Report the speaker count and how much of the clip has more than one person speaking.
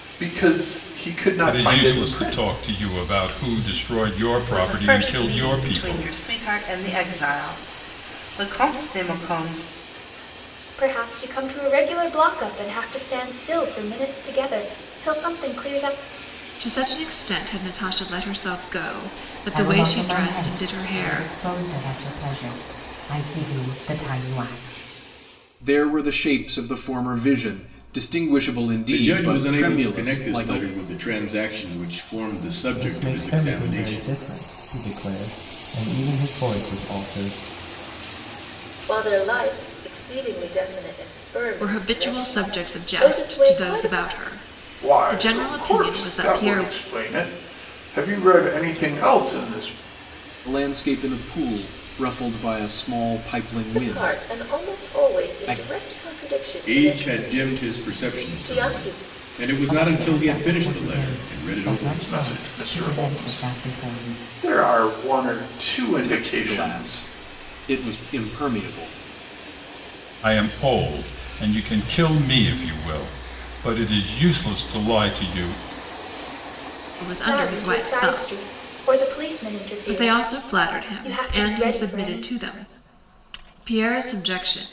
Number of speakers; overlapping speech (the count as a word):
ten, about 30%